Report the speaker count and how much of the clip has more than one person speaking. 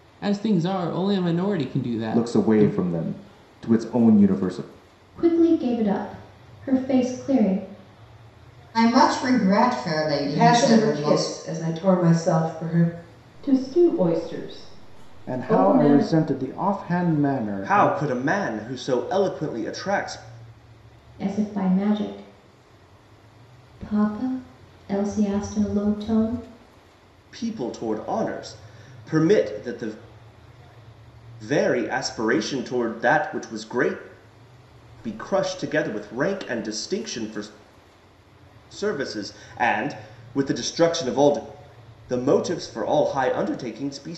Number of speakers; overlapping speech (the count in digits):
8, about 7%